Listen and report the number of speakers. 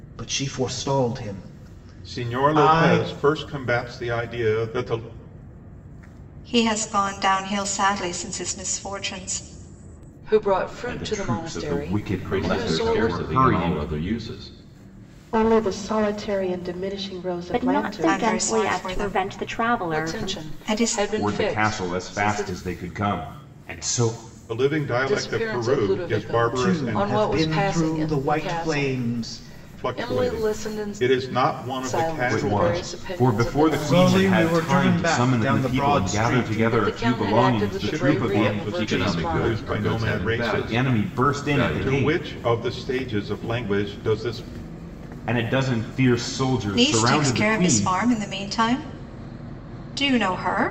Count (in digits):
8